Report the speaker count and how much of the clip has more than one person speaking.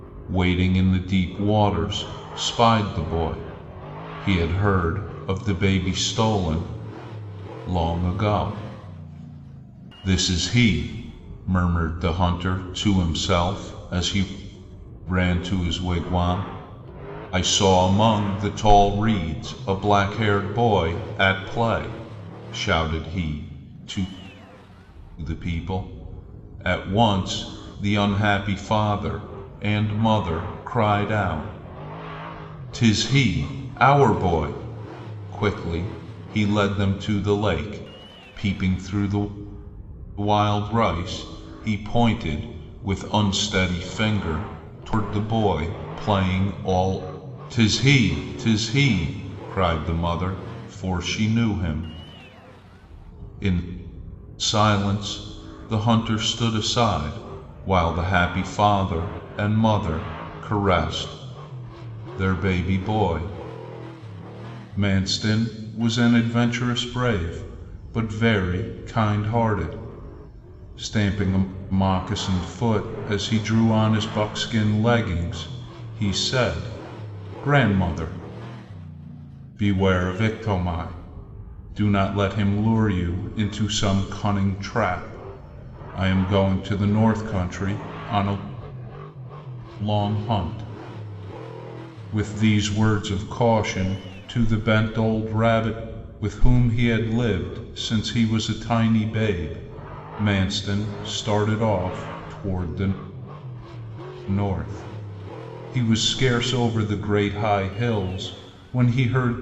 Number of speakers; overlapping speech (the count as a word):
one, no overlap